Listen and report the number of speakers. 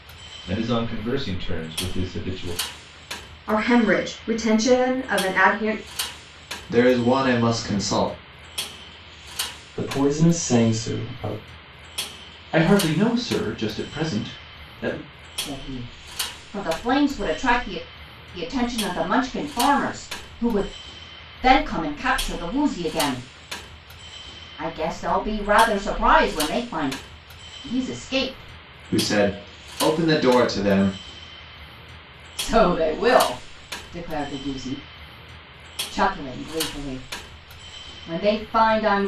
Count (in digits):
6